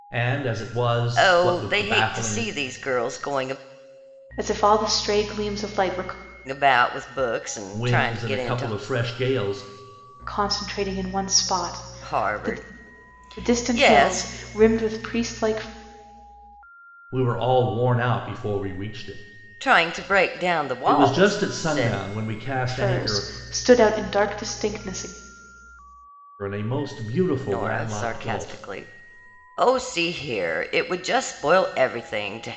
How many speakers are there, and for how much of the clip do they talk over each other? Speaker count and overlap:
three, about 21%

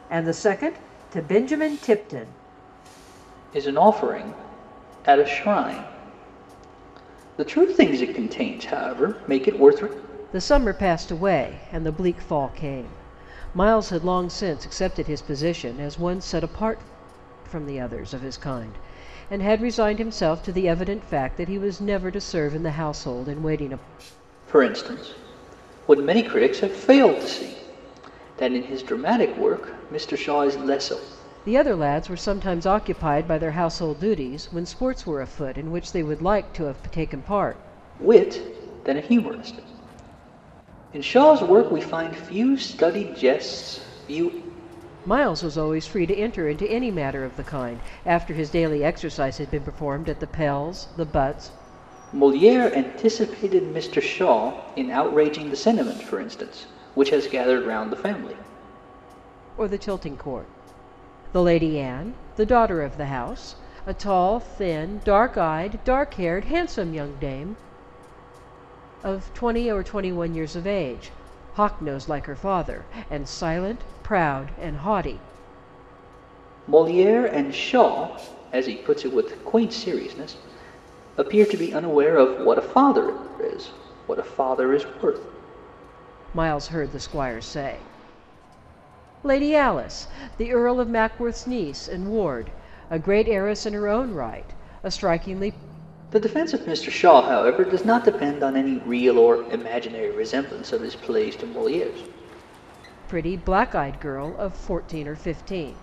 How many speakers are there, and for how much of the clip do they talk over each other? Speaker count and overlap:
two, no overlap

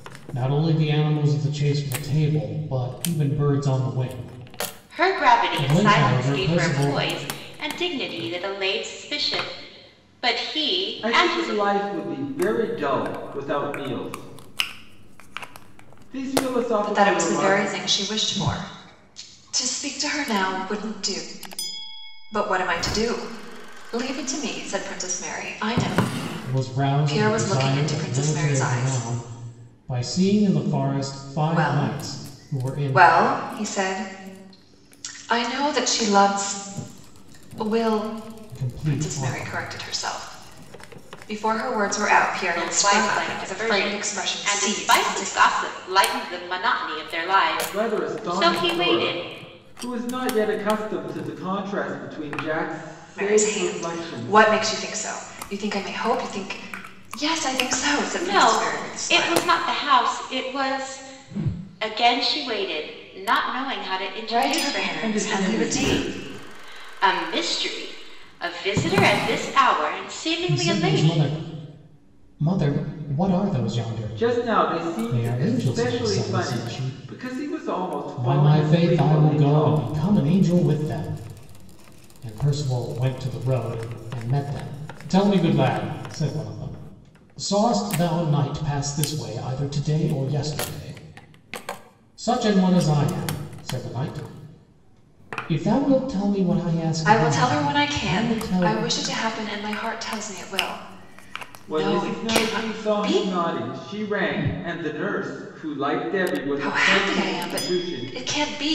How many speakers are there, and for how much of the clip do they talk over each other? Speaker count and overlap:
four, about 26%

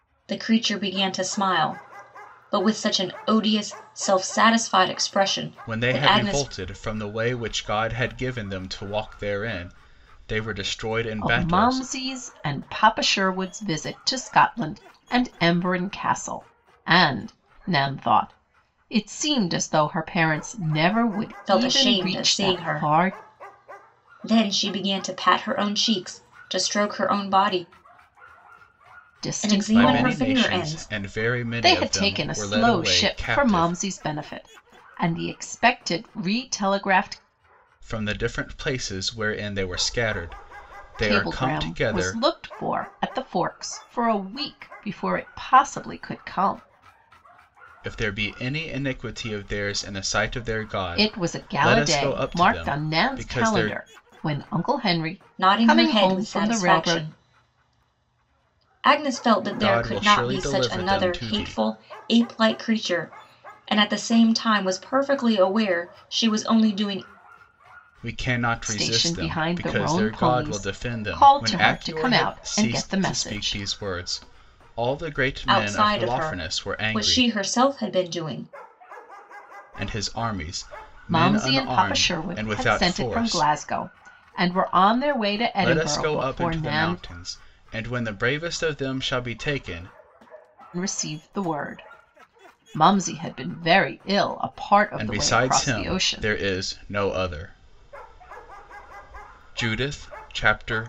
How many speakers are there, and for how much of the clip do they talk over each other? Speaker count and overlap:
three, about 27%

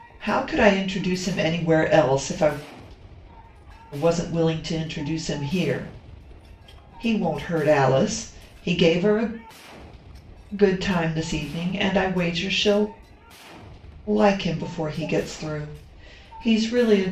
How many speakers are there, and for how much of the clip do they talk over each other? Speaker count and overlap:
one, no overlap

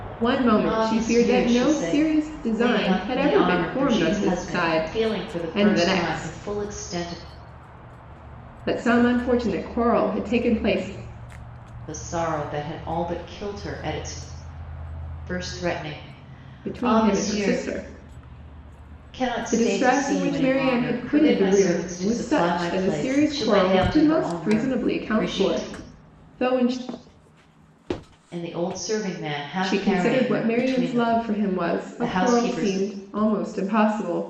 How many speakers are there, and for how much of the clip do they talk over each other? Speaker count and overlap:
two, about 46%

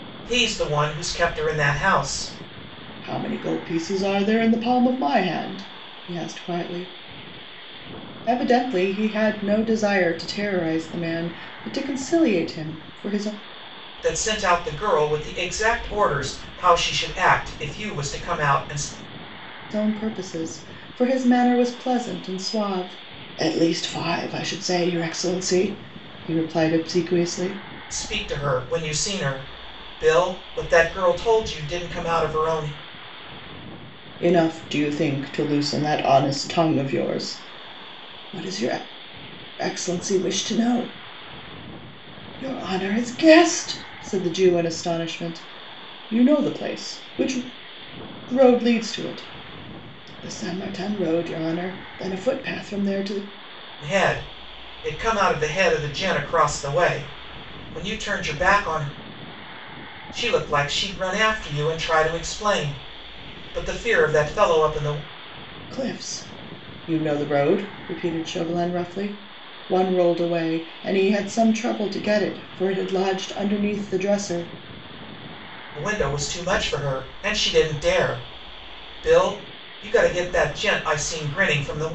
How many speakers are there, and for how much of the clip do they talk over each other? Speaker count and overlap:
two, no overlap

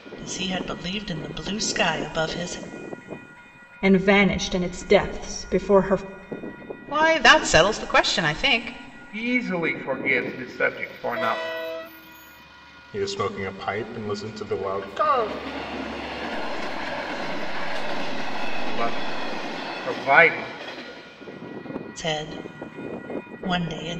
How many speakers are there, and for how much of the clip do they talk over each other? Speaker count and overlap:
six, no overlap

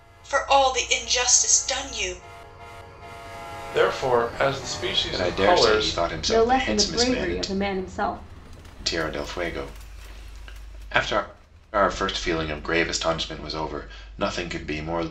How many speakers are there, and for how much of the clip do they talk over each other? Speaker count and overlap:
four, about 14%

